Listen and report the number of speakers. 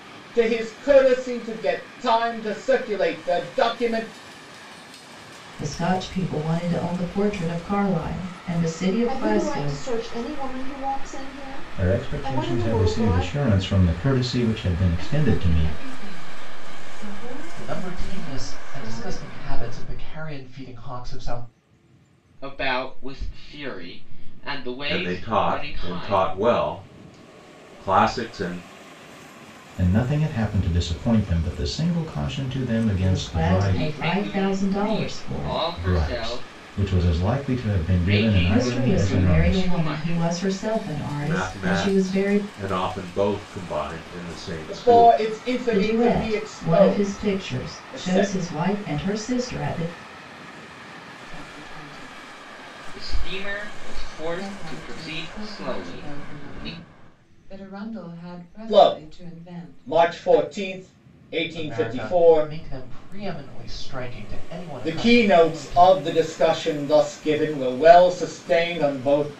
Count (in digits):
8